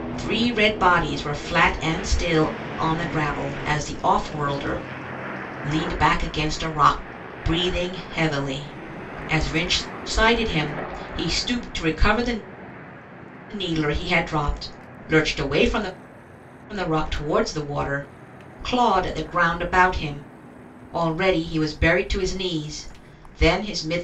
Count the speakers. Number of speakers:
1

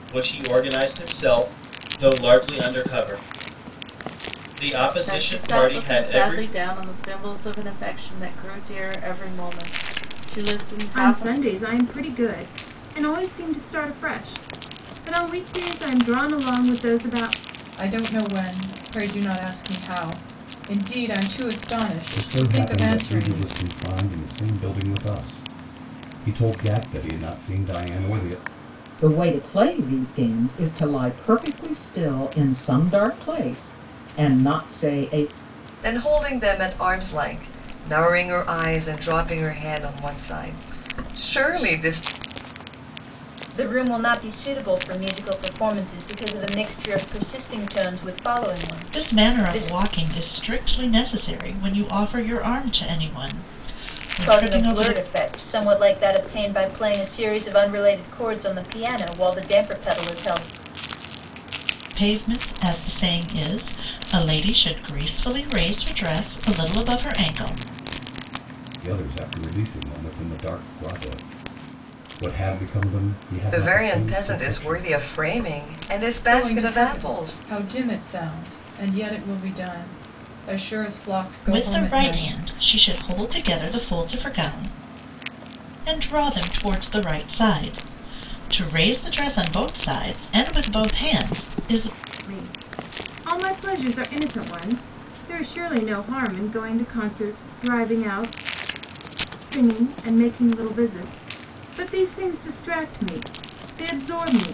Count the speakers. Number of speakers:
9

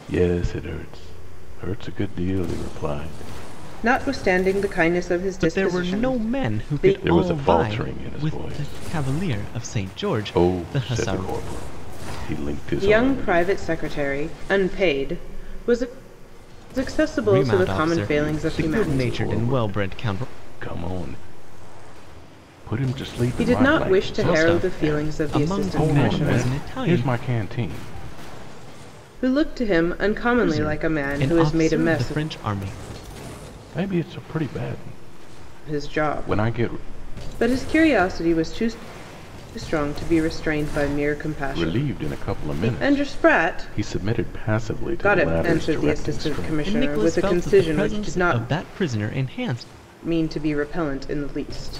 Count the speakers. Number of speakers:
3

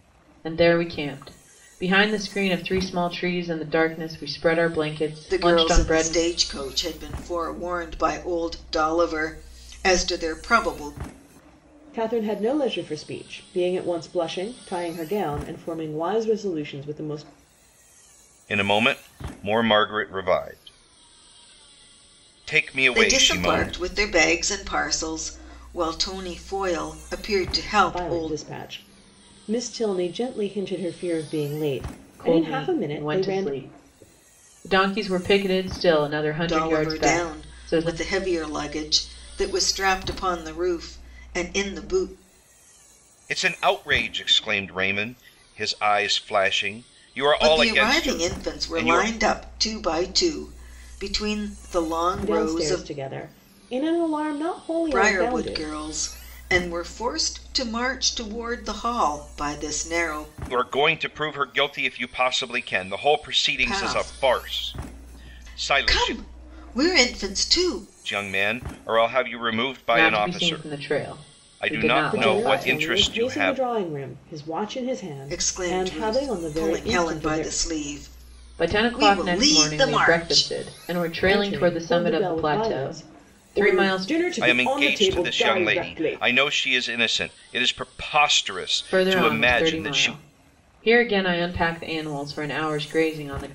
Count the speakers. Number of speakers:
4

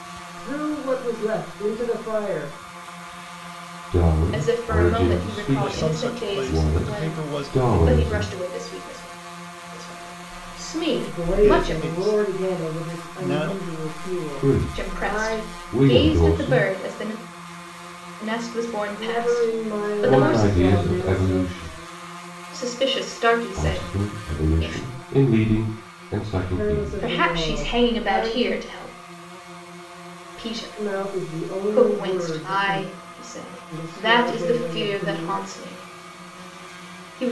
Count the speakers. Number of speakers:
4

